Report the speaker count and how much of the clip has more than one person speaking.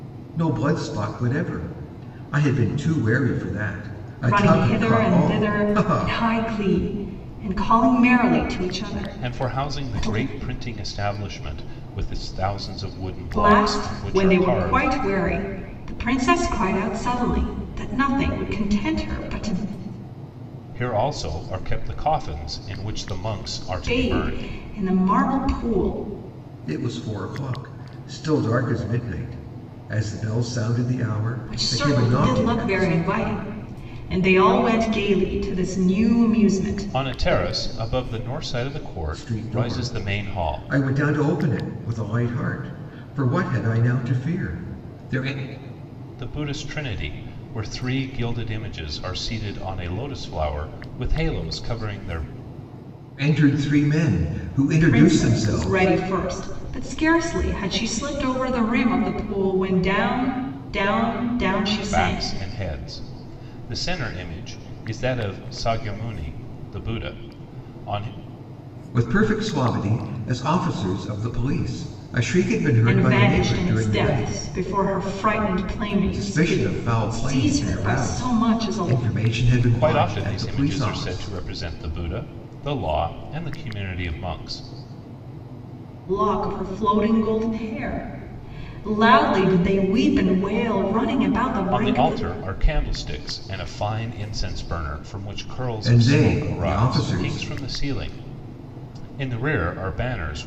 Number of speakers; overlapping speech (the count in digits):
3, about 19%